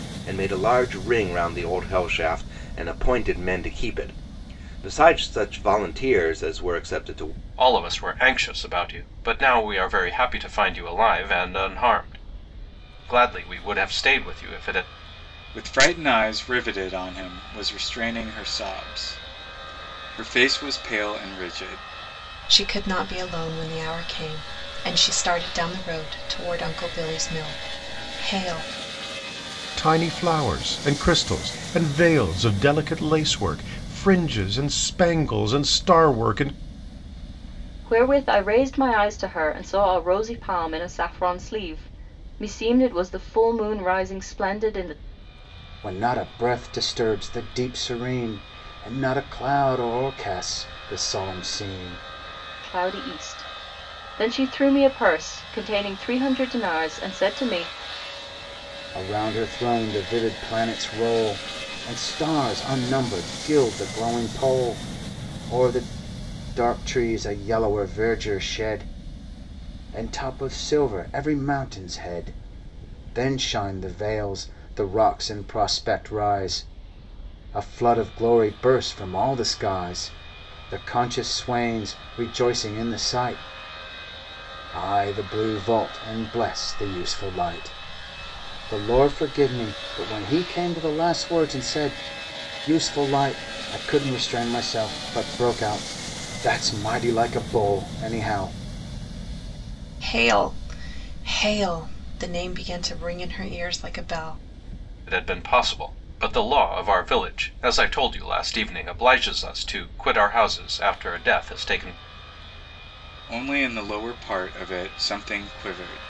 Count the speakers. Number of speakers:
7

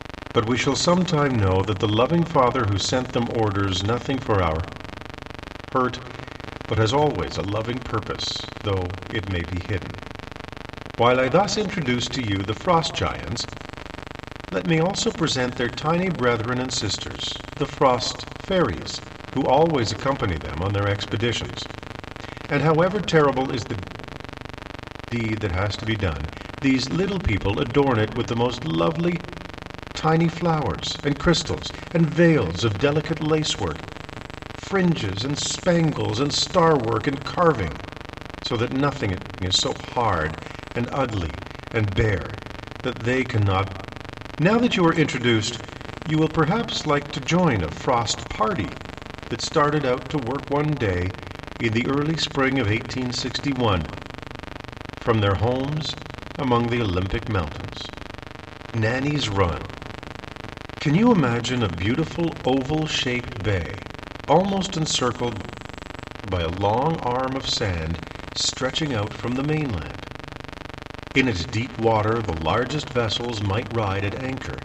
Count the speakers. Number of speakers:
1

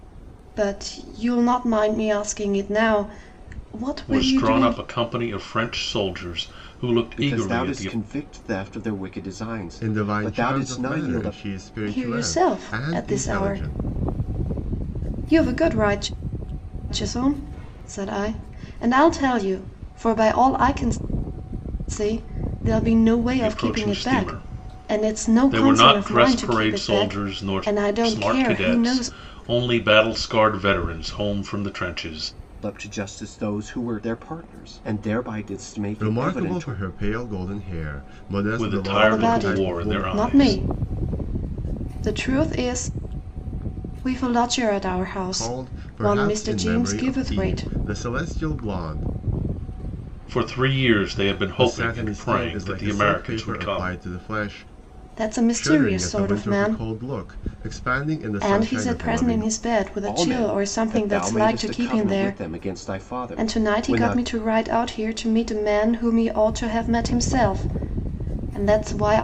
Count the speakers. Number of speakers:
4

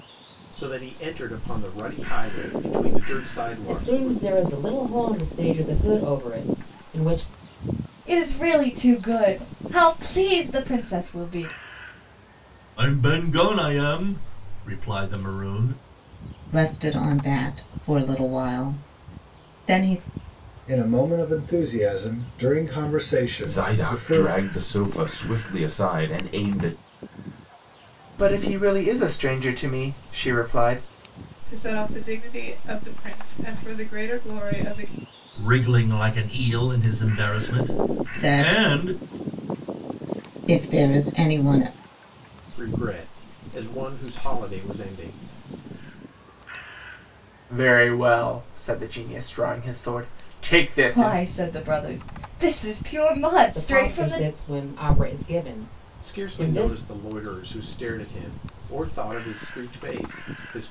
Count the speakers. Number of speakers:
9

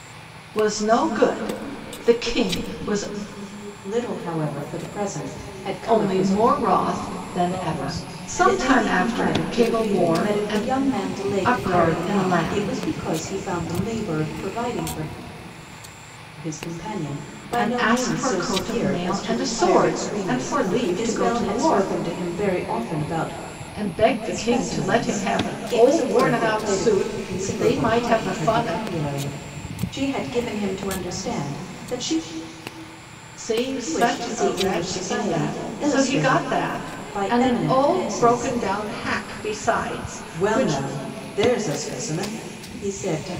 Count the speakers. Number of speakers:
2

